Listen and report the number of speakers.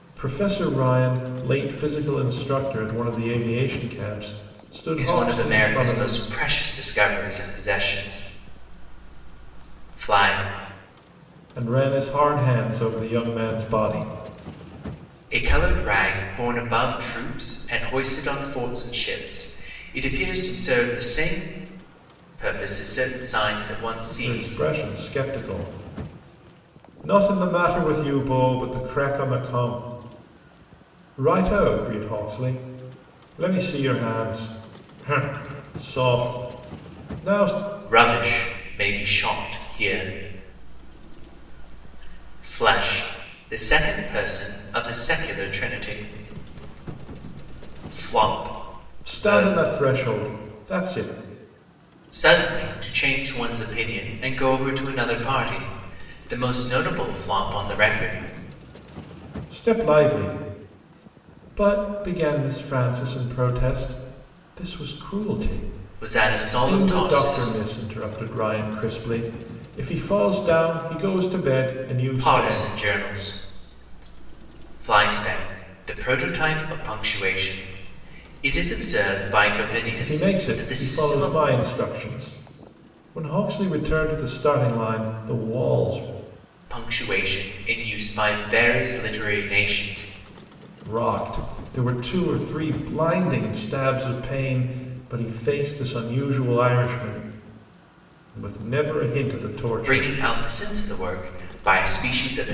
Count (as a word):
two